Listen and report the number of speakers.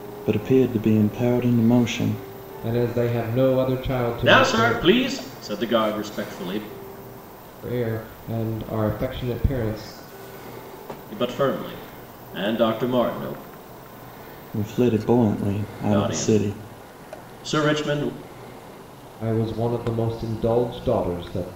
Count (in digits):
3